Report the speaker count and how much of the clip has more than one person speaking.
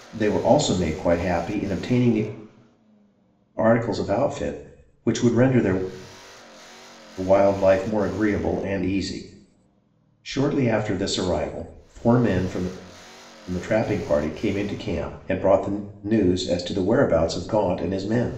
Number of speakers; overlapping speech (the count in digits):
1, no overlap